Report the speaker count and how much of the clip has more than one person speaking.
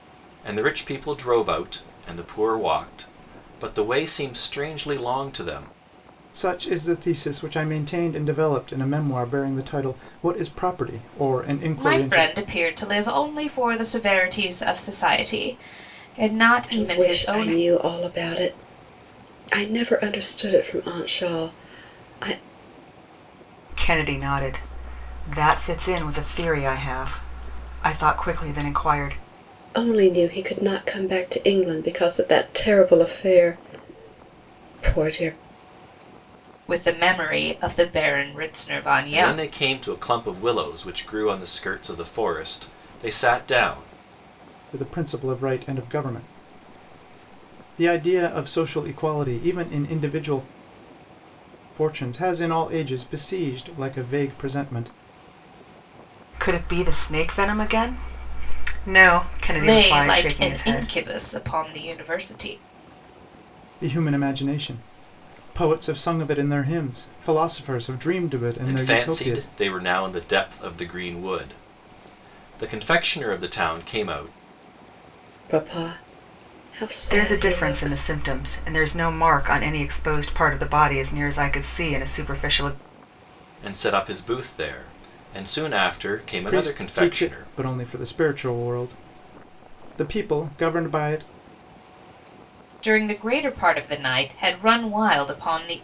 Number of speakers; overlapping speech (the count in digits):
5, about 7%